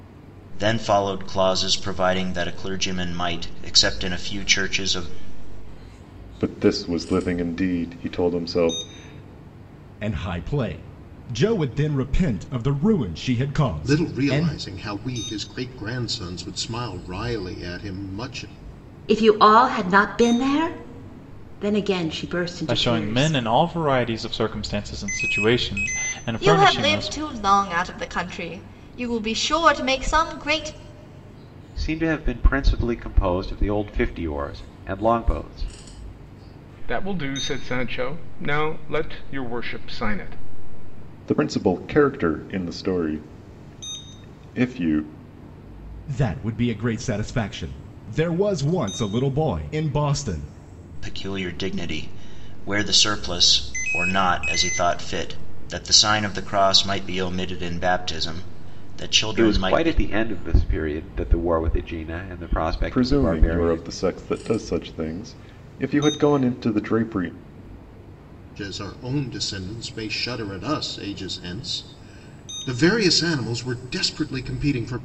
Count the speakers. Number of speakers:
9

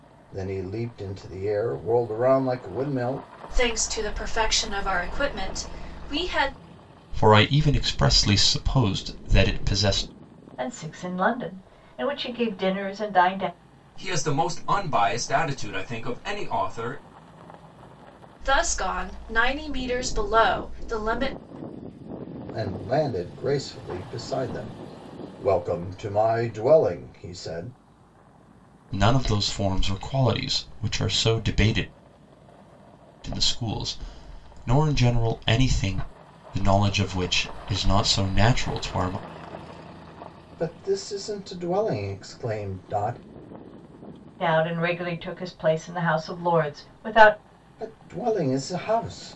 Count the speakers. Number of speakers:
5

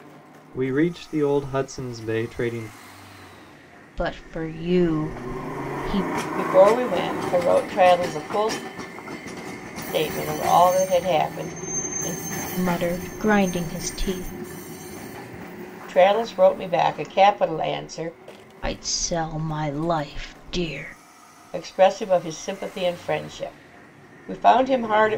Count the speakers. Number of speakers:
3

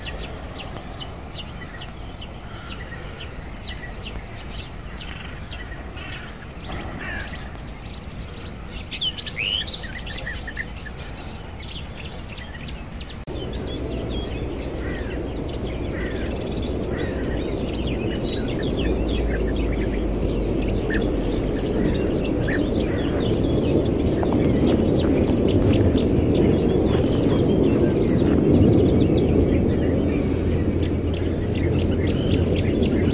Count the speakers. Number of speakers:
0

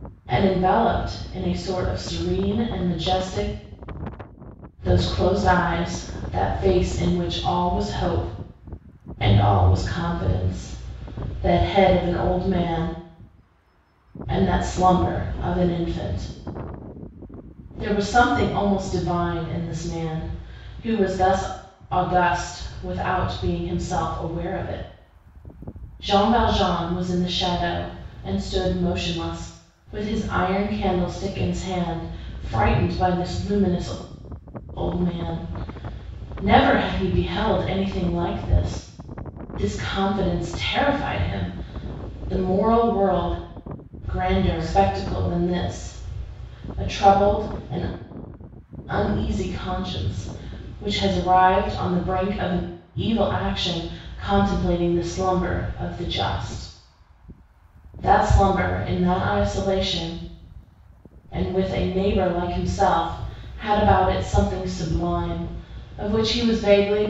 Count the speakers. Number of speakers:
1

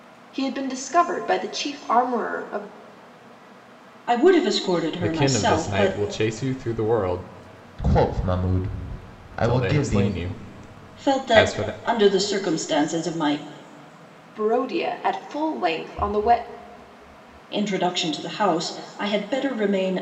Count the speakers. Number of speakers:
4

